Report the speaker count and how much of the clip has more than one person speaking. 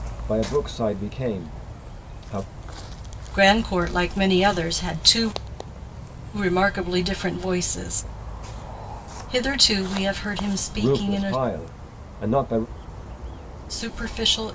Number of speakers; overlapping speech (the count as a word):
two, about 4%